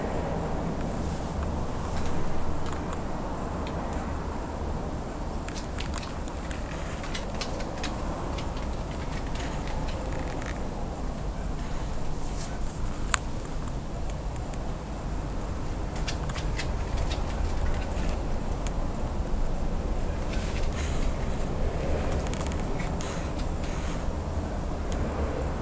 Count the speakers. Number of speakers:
zero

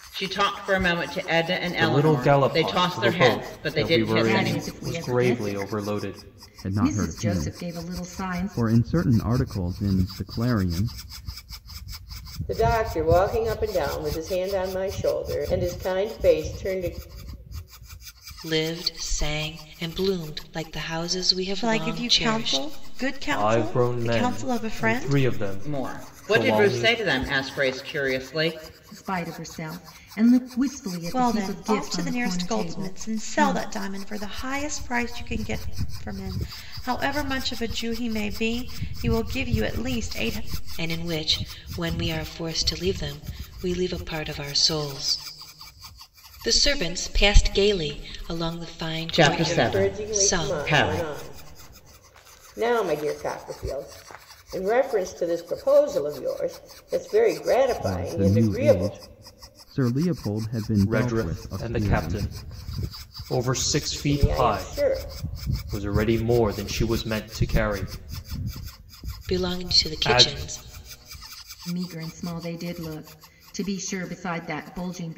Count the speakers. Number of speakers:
seven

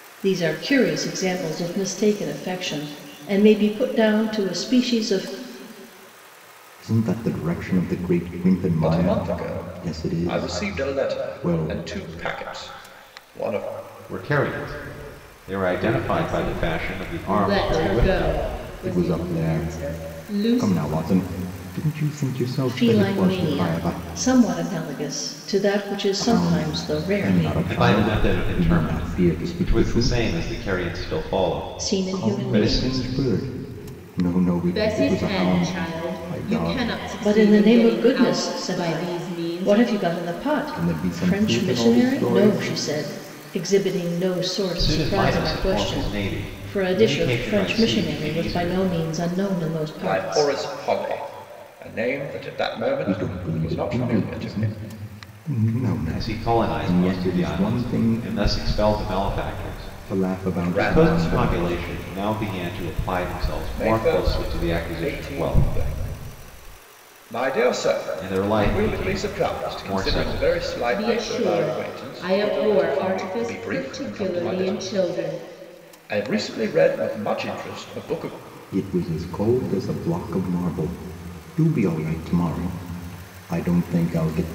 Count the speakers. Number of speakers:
five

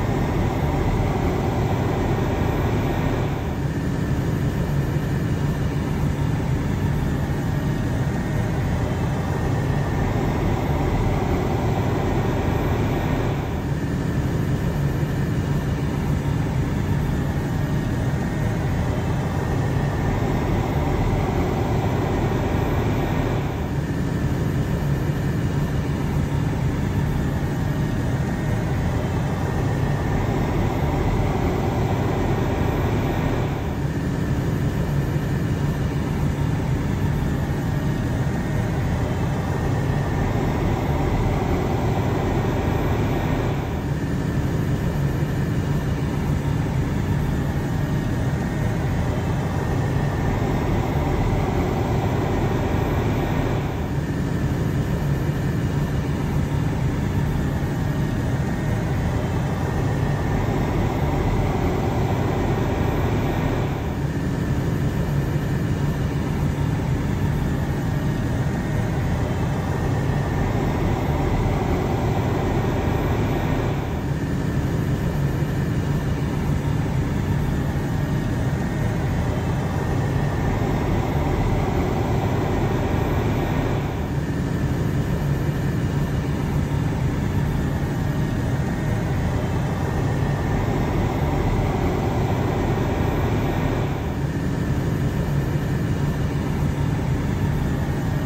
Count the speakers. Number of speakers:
zero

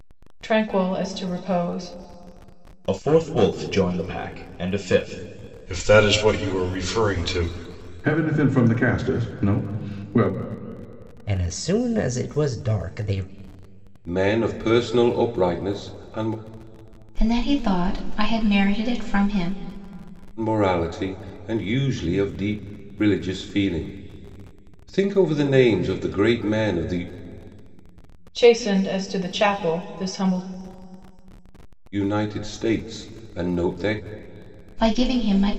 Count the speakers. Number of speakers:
seven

